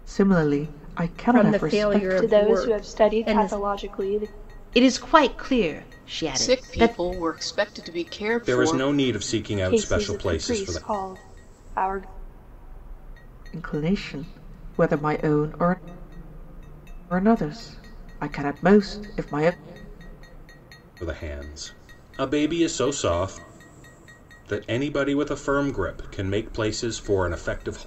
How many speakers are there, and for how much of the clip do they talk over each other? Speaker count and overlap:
6, about 17%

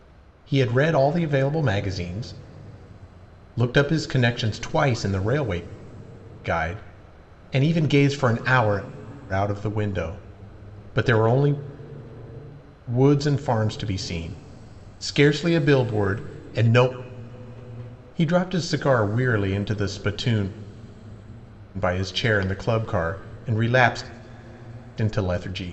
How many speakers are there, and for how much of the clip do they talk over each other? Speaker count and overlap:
1, no overlap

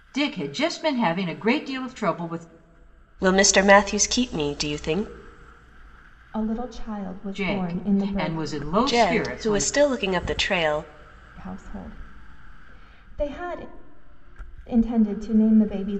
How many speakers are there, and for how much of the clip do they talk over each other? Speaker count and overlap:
3, about 13%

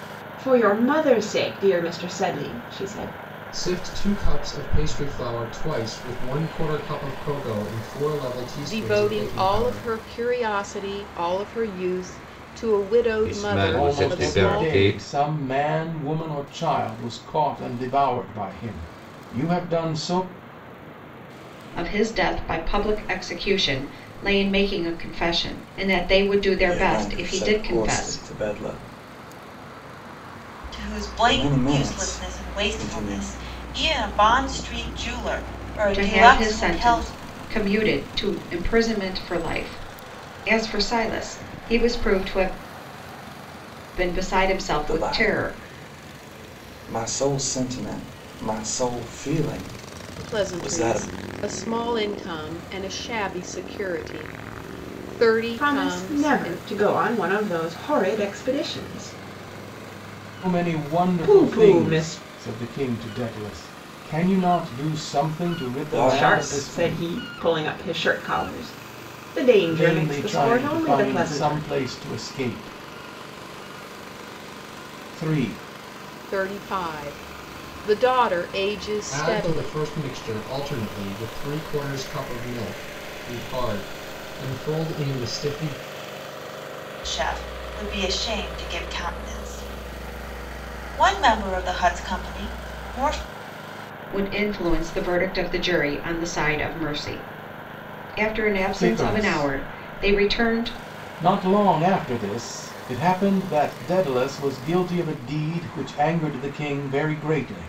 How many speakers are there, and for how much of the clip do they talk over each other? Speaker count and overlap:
8, about 18%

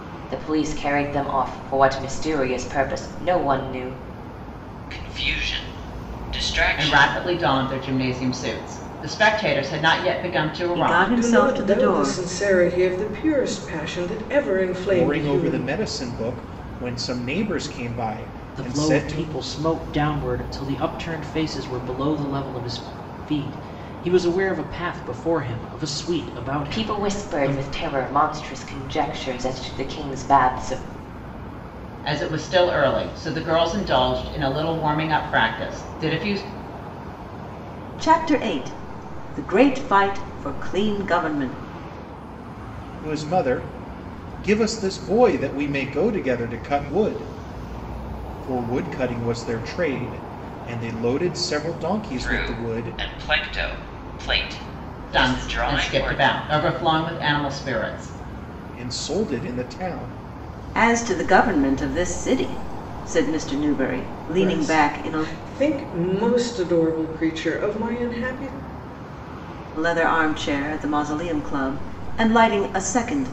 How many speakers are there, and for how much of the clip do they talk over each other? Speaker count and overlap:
7, about 10%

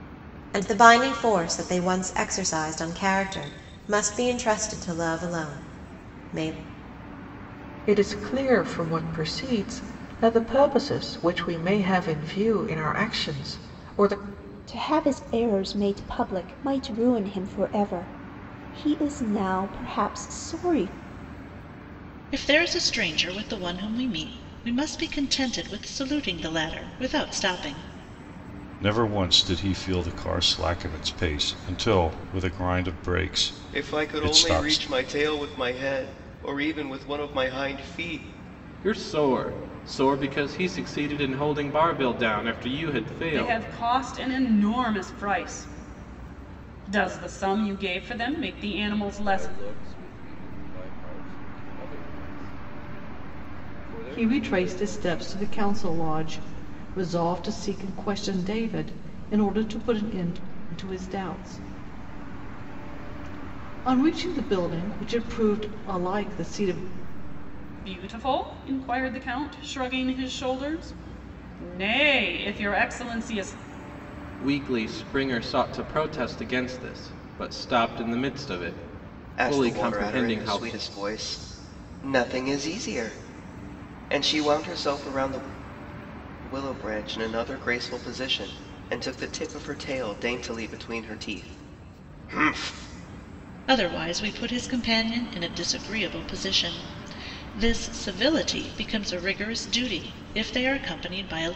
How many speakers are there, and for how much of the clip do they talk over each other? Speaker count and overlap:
10, about 5%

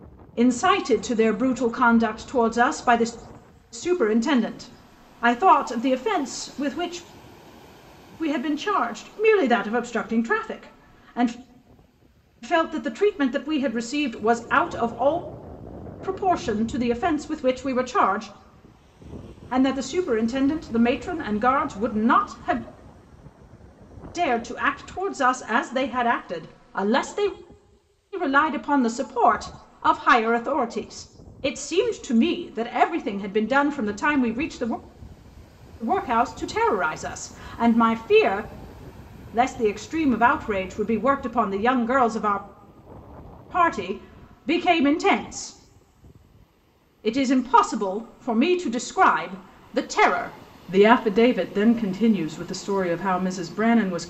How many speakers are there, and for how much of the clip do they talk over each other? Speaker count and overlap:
1, no overlap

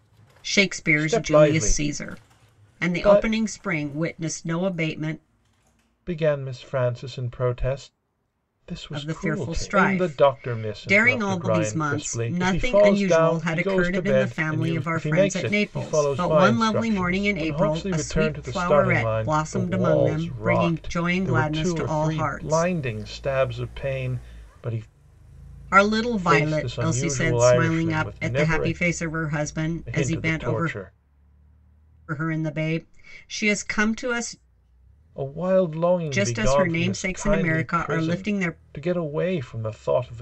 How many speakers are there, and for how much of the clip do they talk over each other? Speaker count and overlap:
2, about 54%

